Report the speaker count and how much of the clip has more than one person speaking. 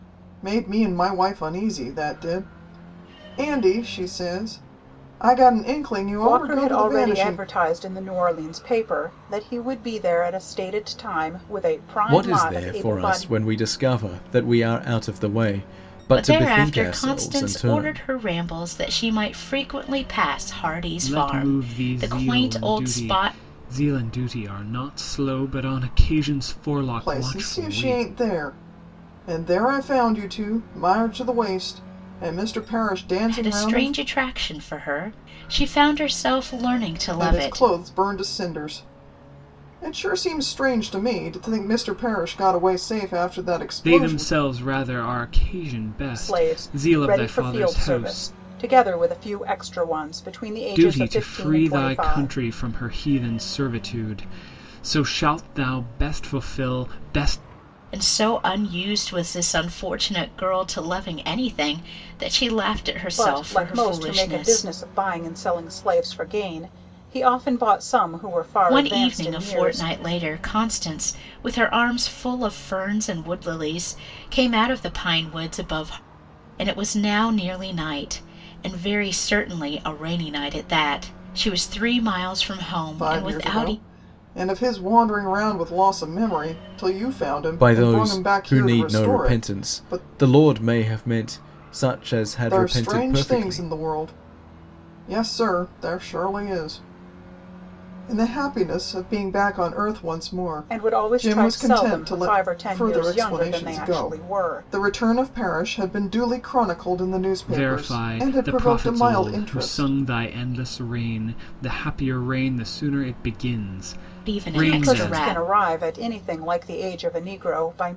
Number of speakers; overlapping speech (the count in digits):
5, about 24%